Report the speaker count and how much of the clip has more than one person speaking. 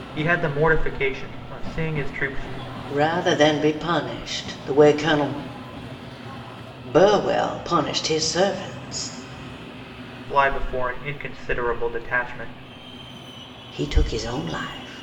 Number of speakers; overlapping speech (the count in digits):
2, no overlap